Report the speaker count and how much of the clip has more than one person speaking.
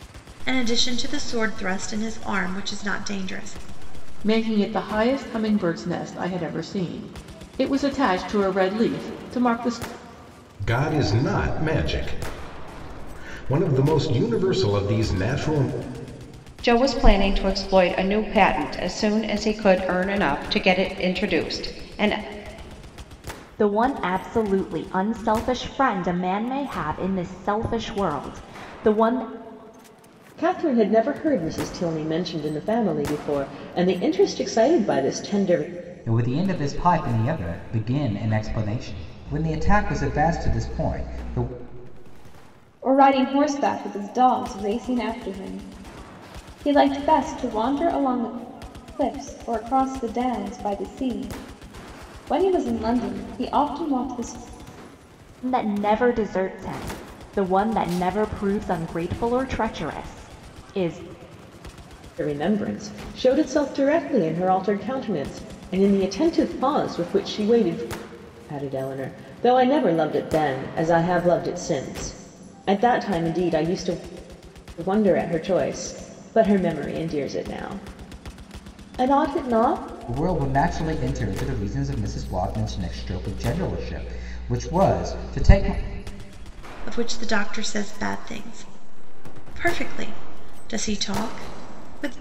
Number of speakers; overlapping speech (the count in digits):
8, no overlap